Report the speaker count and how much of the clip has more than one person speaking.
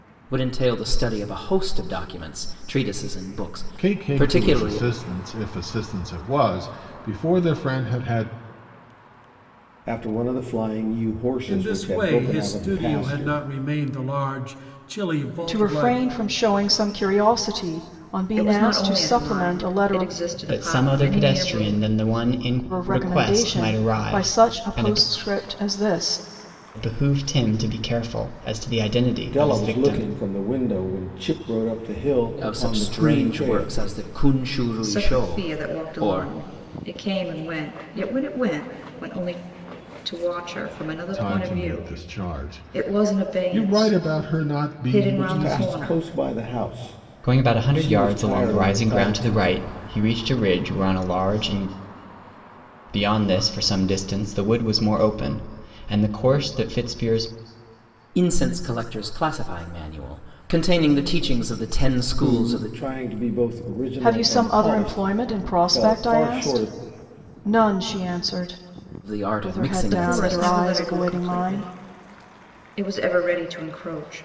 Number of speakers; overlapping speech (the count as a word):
seven, about 35%